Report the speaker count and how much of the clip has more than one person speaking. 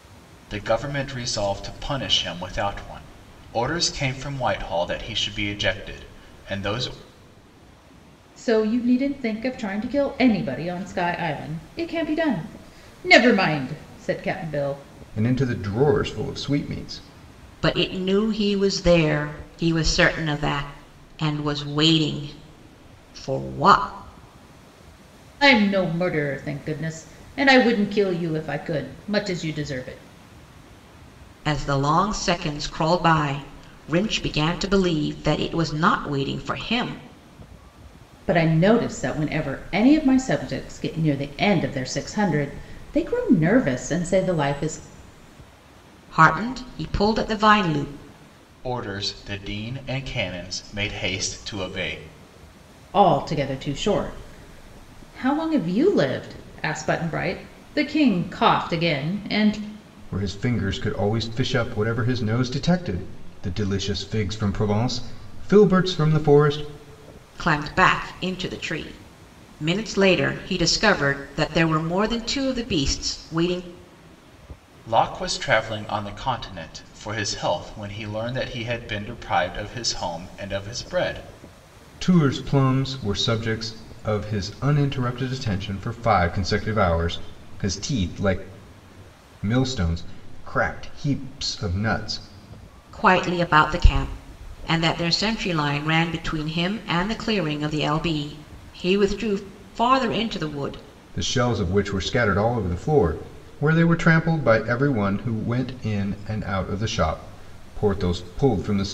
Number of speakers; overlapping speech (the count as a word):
four, no overlap